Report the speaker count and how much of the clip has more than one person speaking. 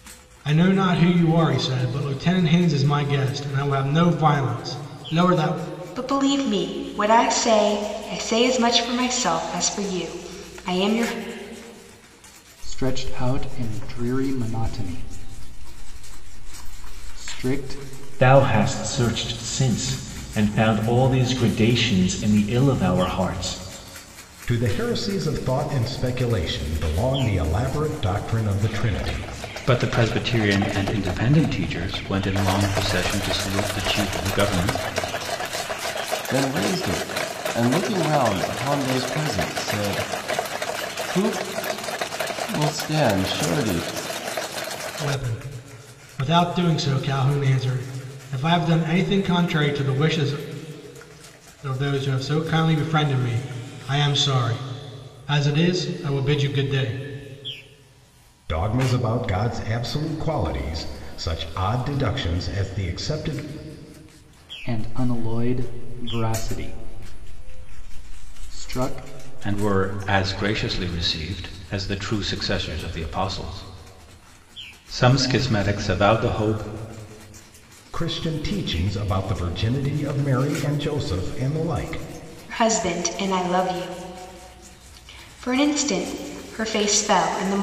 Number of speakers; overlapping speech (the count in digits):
7, no overlap